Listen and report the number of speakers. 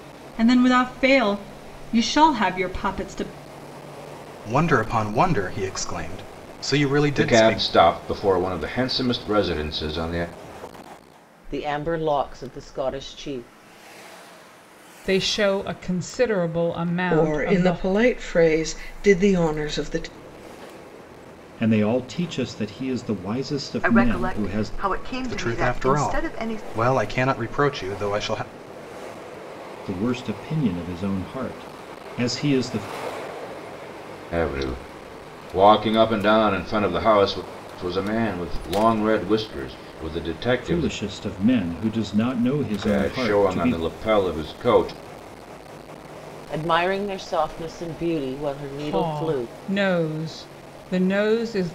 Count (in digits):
8